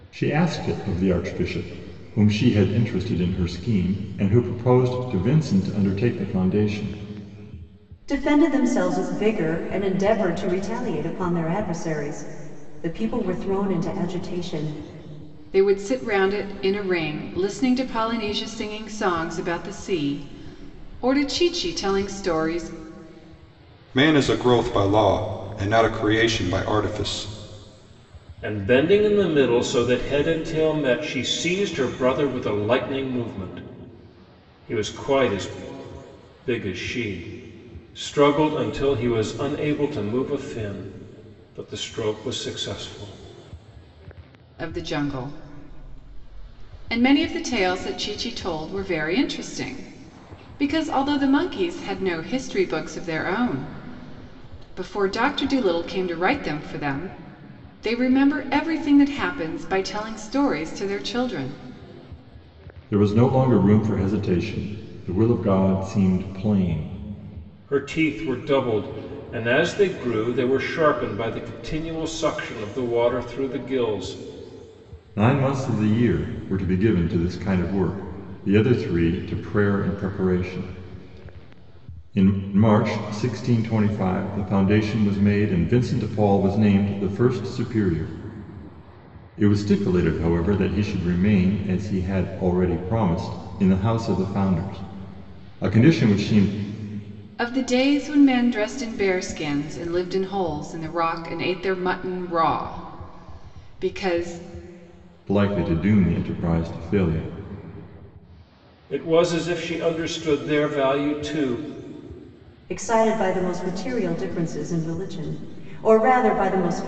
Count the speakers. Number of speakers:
5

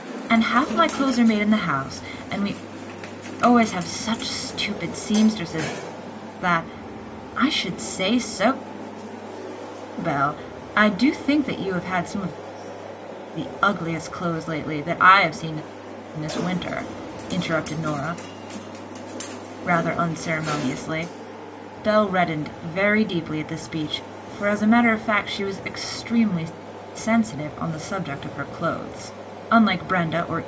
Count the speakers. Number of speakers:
1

